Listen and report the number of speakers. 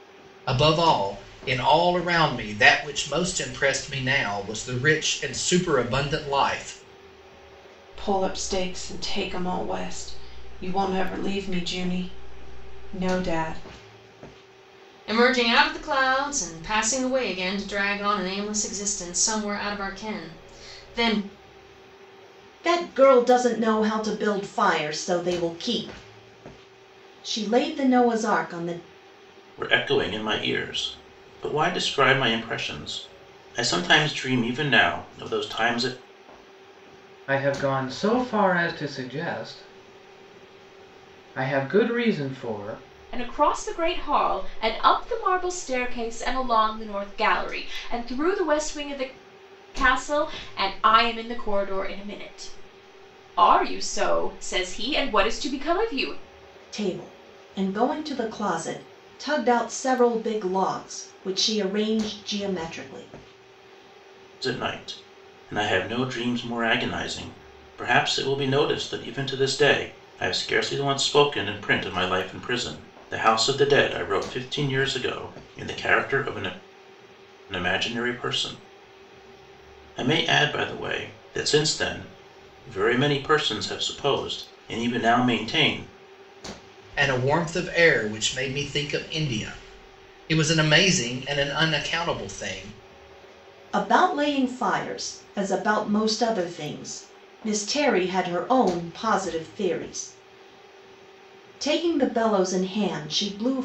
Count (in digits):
7